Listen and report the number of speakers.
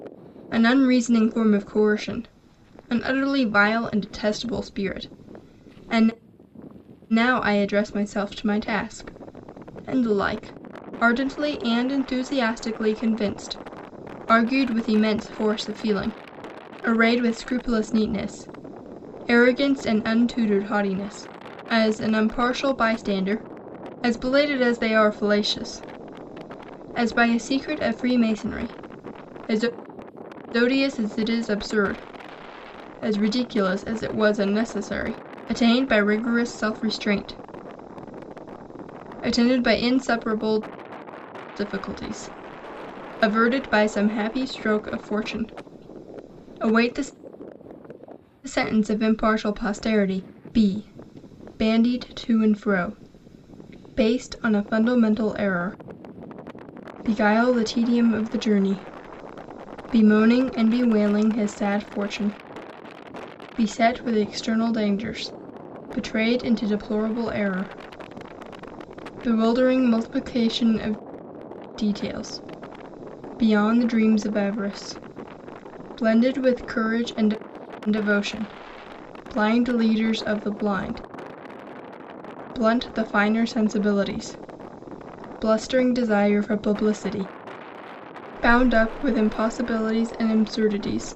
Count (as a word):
one